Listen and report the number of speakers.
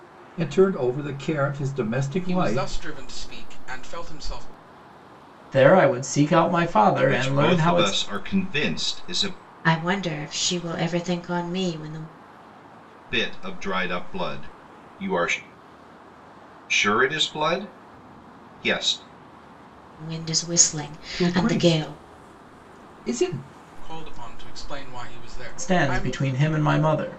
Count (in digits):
5